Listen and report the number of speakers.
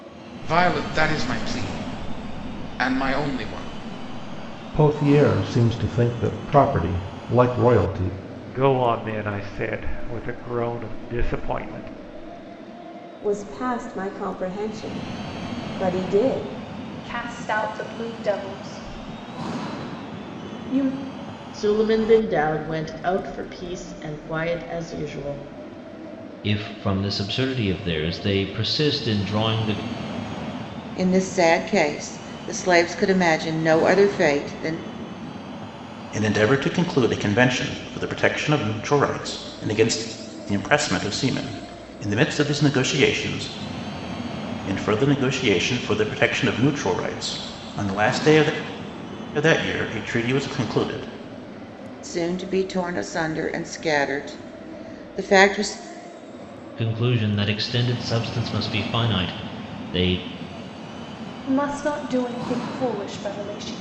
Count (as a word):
nine